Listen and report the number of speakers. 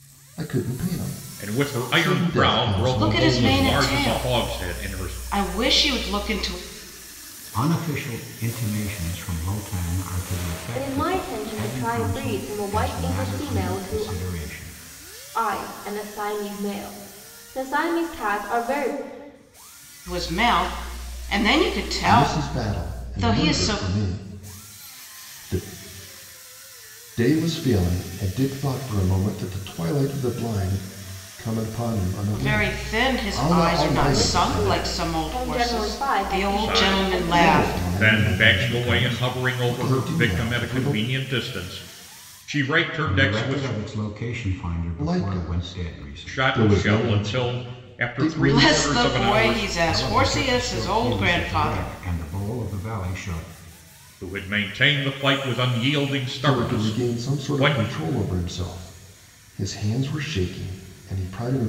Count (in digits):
5